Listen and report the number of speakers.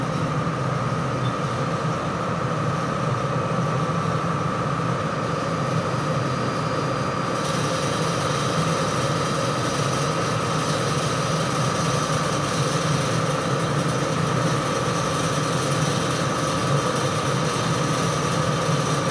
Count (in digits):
0